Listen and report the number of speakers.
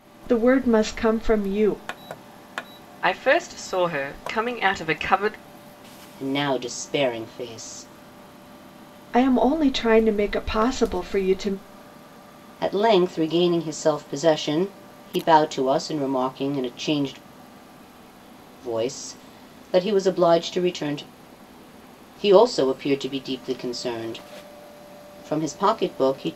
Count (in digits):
3